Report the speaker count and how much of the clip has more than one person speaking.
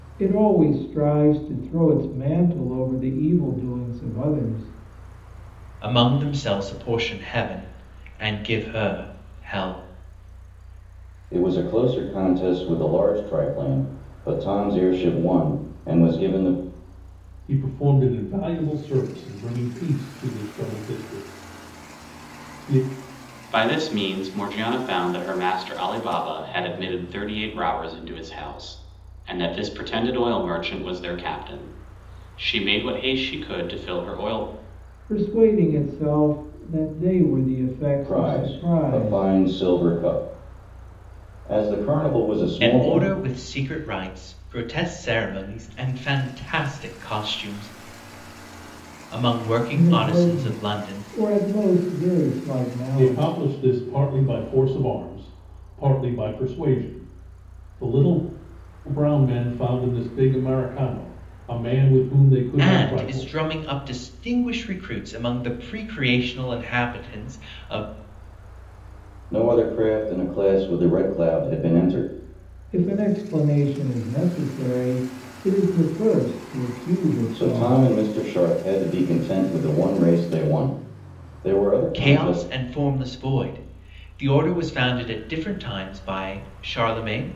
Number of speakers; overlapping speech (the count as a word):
five, about 7%